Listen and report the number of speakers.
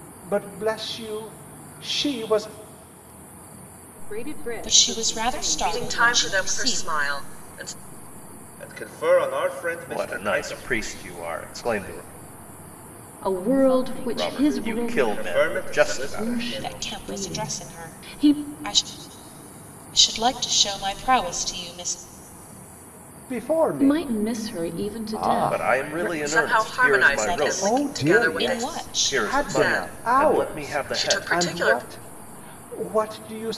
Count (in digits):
7